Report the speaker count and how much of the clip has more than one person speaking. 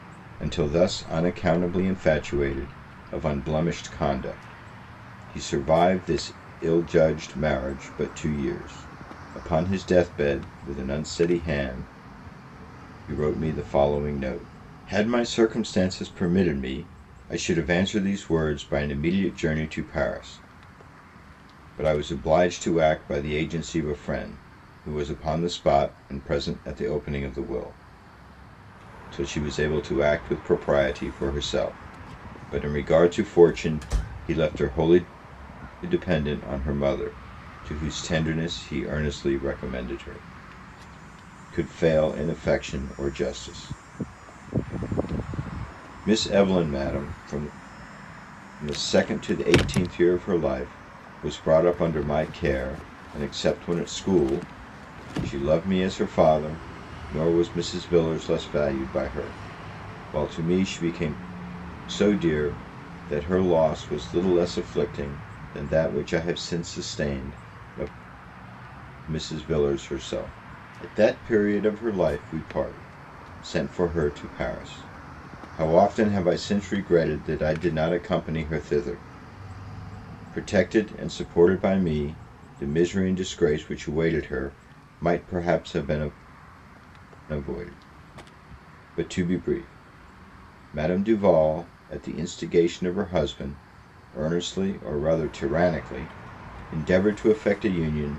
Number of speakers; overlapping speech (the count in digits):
1, no overlap